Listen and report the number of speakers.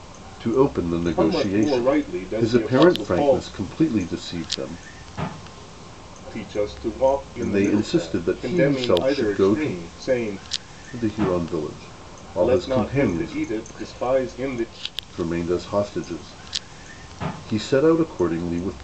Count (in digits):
2